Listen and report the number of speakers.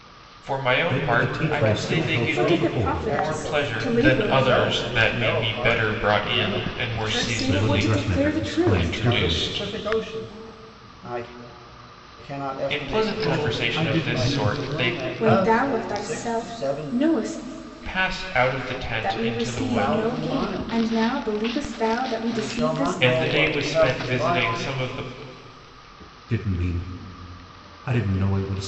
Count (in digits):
4